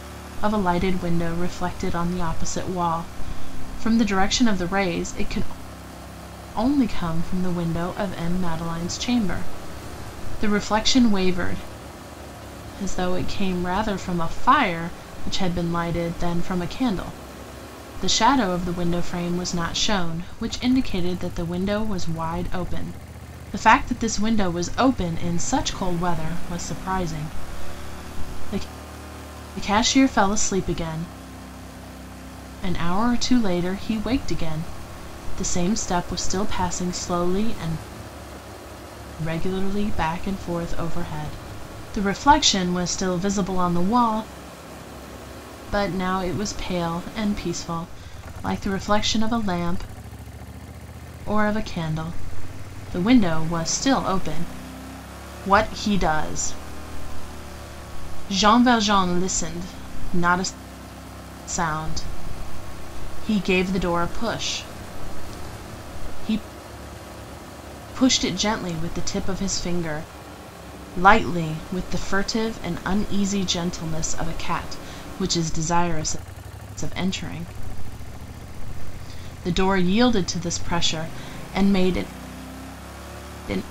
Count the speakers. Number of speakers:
one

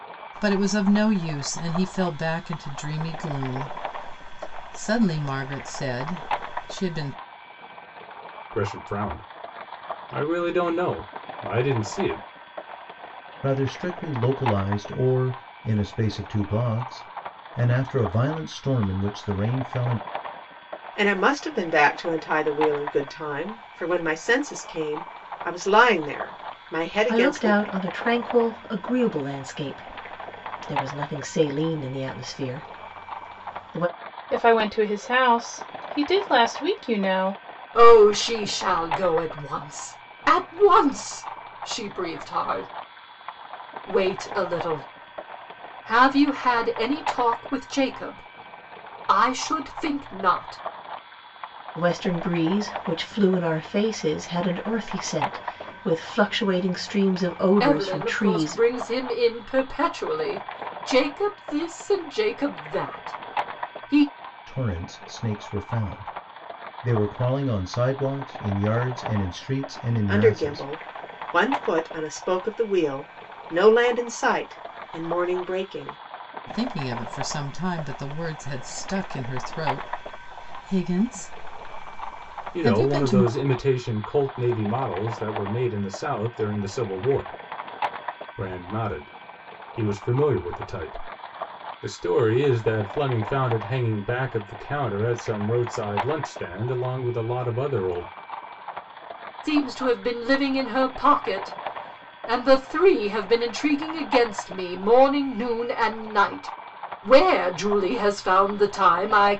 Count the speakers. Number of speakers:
seven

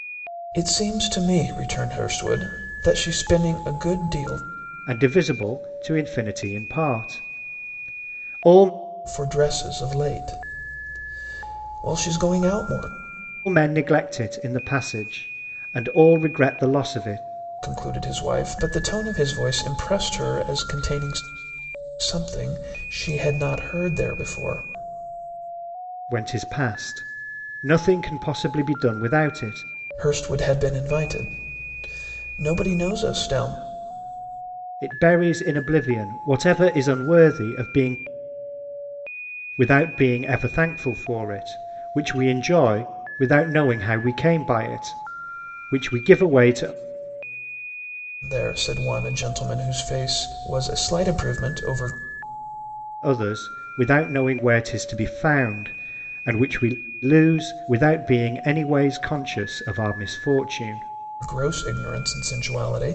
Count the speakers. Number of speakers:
two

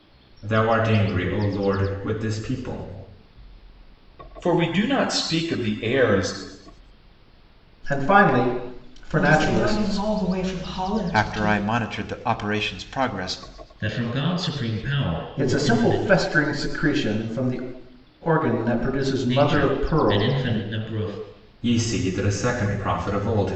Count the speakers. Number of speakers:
six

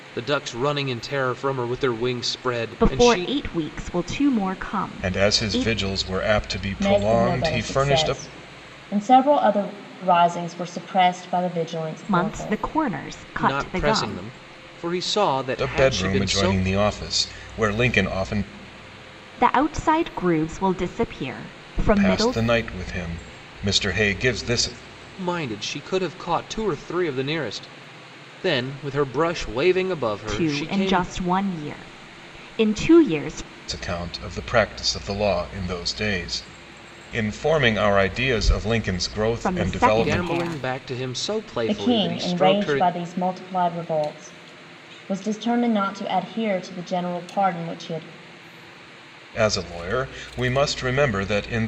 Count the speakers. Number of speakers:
four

